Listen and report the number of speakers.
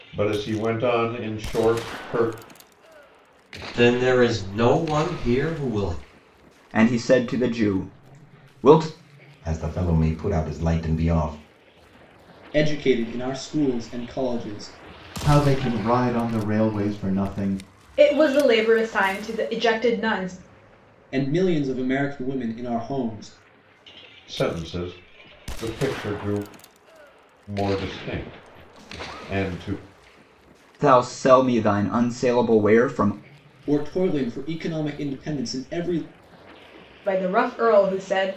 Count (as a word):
seven